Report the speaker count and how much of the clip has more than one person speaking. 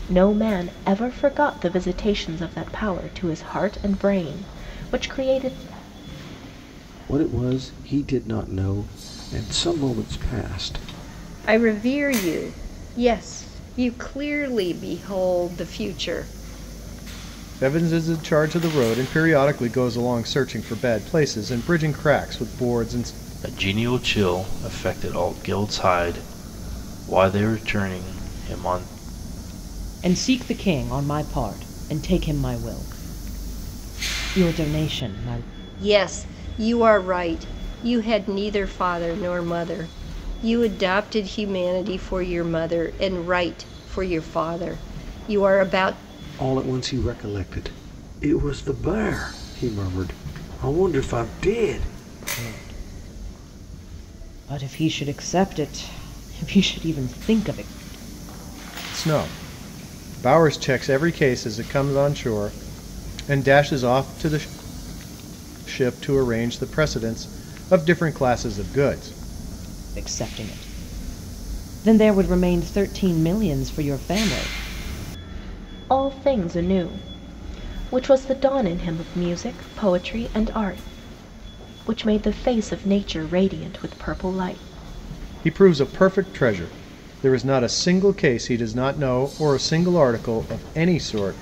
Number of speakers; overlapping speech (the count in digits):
6, no overlap